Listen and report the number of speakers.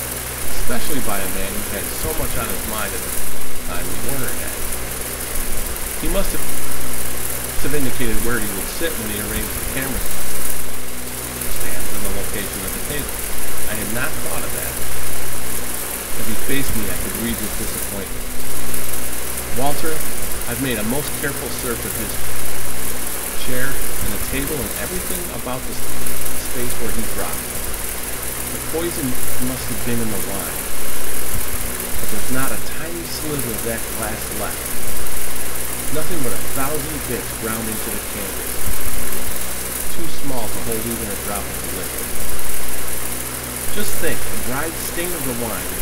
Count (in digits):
1